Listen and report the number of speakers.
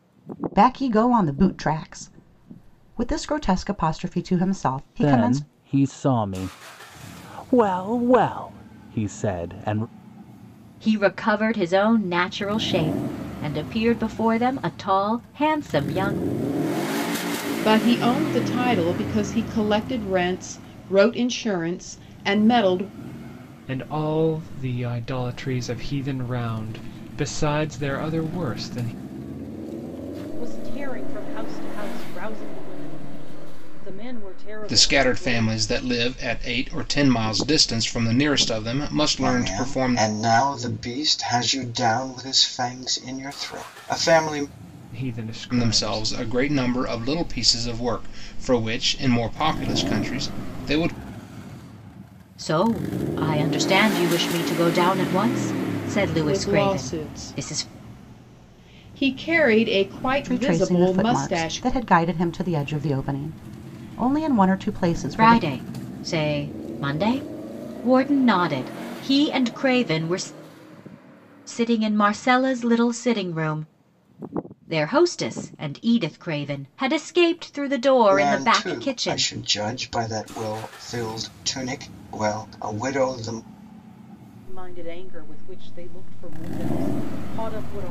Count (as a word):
eight